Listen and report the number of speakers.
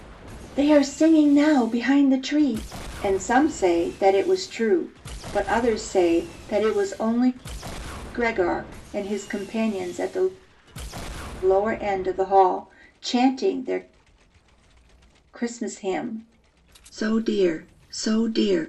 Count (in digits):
1